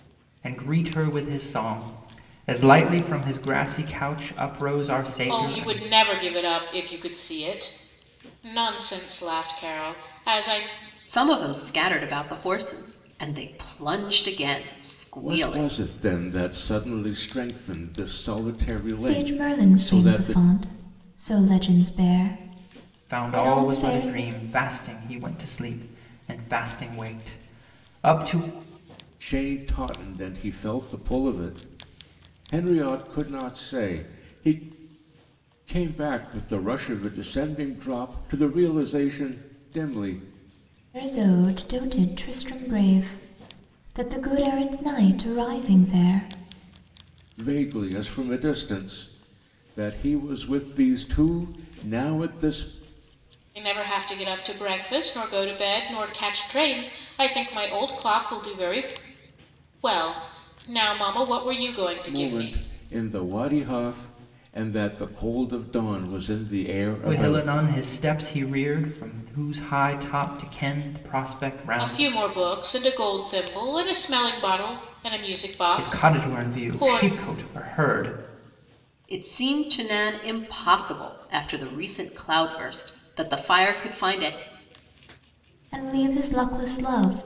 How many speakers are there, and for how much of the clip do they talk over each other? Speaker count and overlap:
five, about 7%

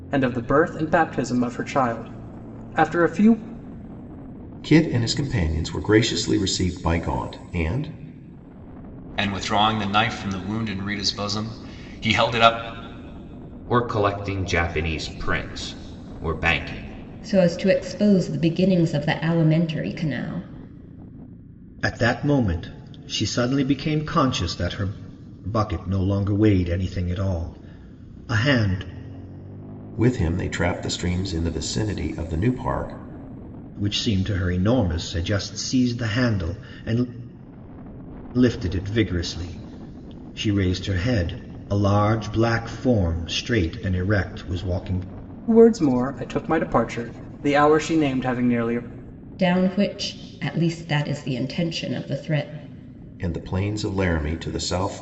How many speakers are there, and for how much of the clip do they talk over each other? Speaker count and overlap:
six, no overlap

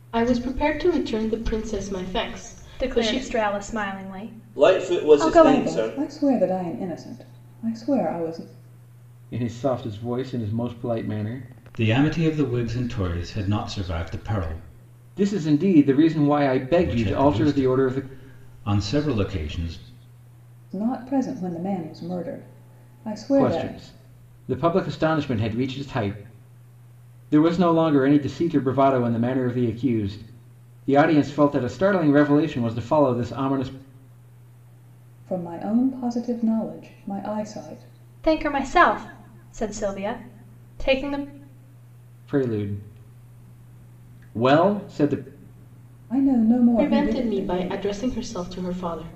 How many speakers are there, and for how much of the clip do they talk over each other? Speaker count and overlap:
six, about 10%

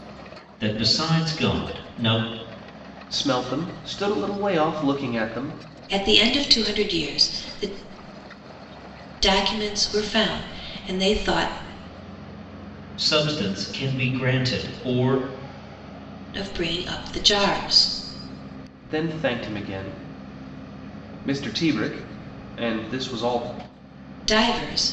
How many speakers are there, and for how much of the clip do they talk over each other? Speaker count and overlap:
three, no overlap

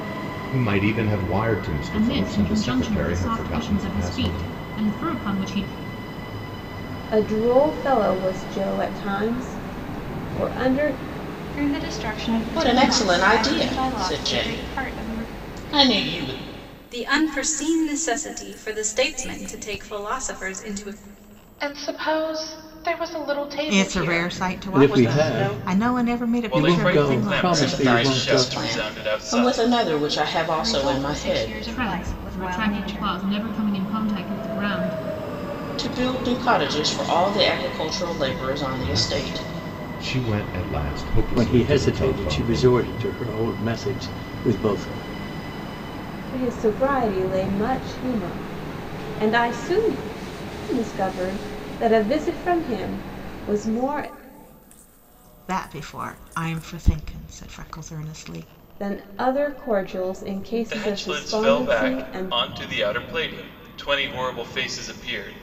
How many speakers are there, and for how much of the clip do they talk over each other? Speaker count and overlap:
ten, about 27%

